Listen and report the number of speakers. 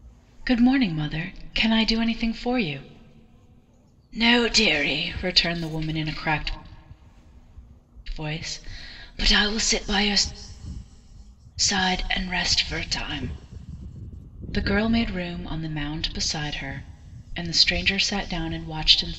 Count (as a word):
one